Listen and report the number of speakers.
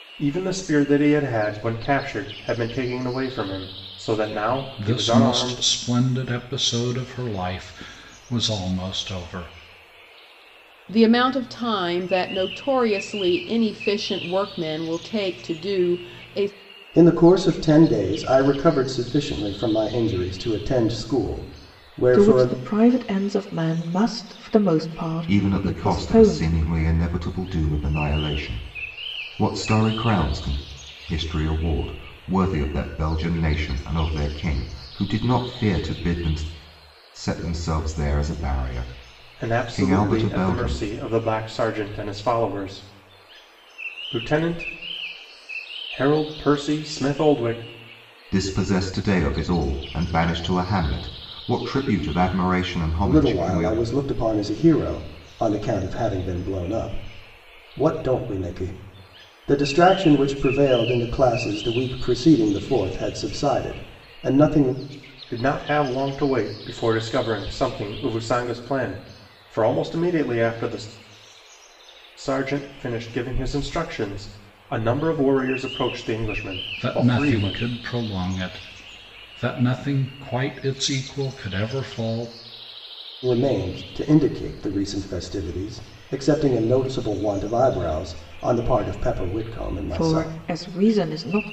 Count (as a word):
six